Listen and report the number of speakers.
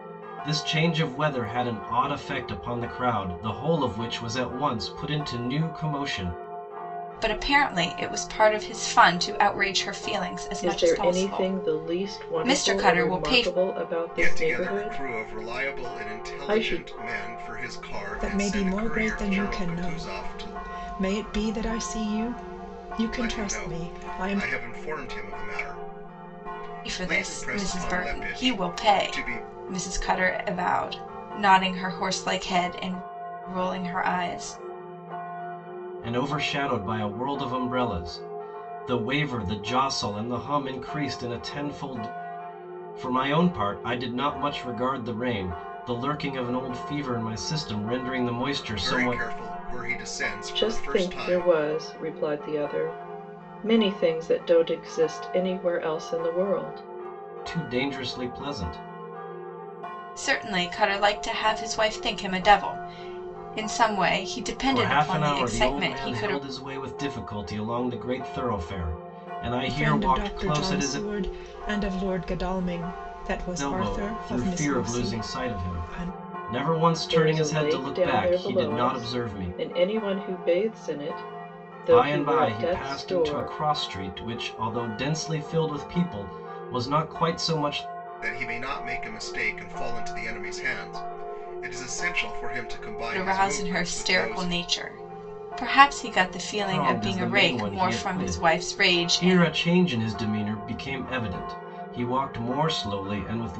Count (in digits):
5